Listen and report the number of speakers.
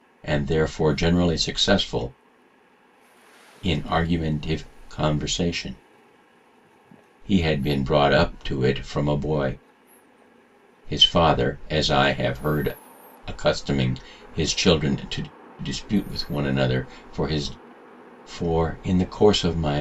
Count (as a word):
one